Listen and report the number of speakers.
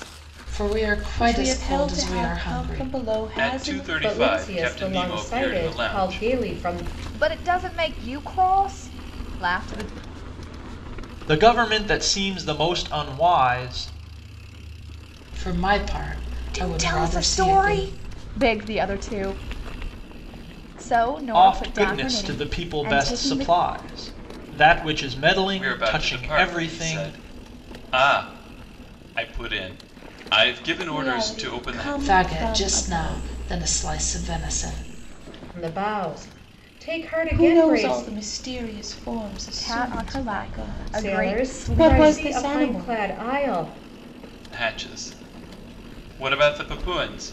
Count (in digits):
6